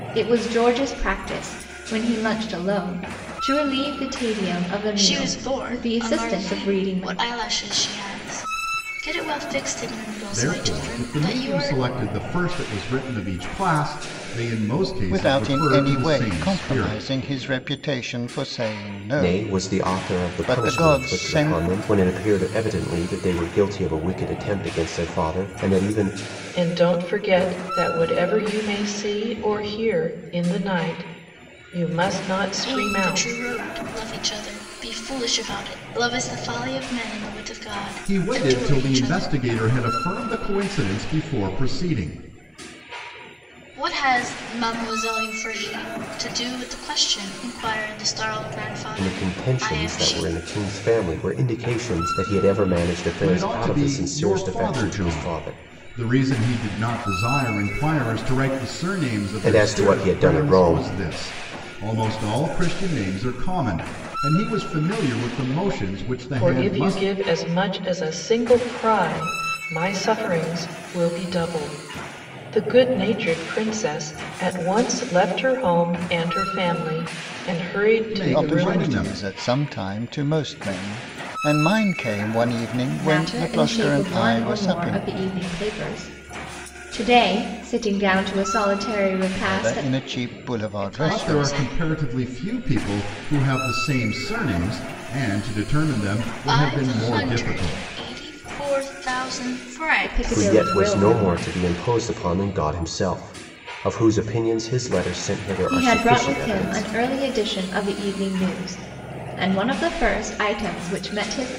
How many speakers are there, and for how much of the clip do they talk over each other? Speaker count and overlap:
6, about 23%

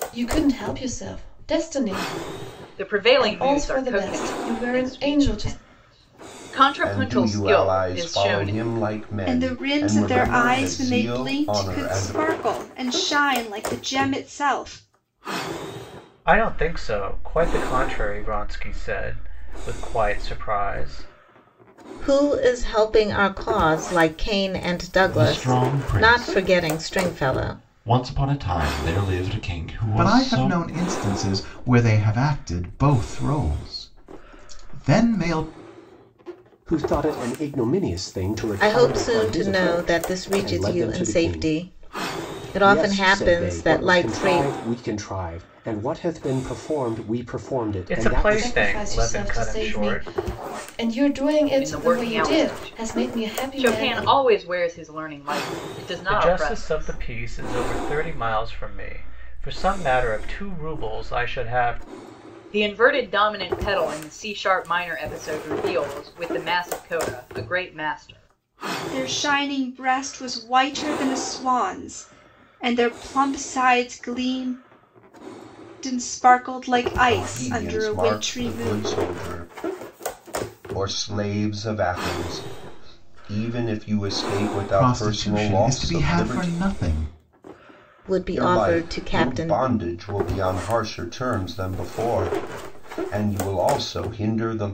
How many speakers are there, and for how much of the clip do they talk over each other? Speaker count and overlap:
9, about 28%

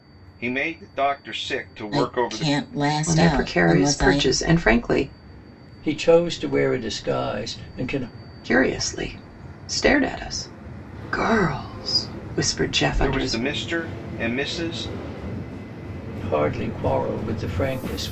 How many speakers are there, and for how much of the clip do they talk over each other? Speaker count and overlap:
4, about 13%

